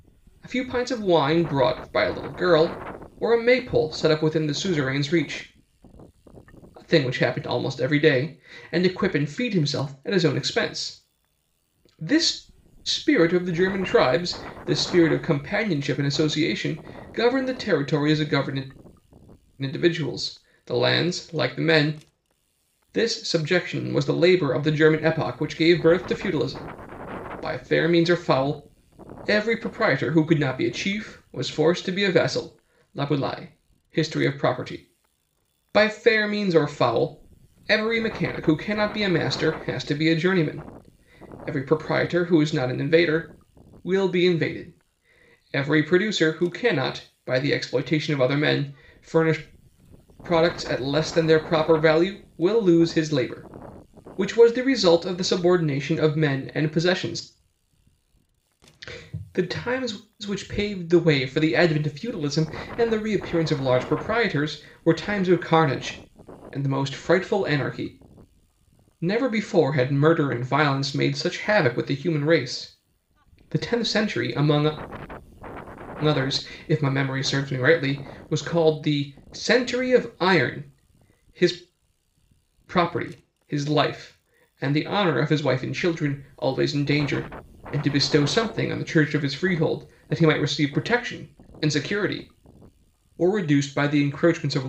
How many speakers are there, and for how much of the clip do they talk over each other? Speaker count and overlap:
1, no overlap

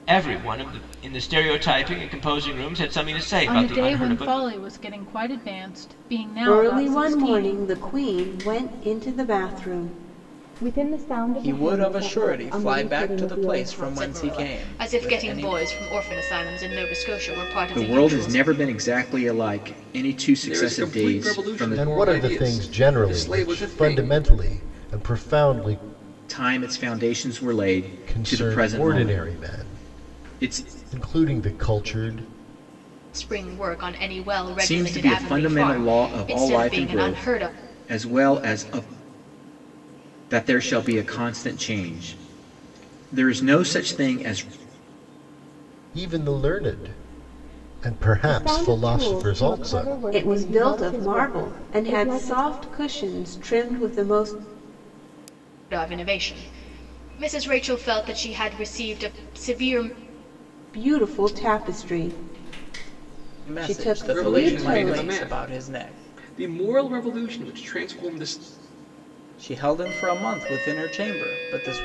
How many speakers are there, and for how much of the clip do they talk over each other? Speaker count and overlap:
9, about 32%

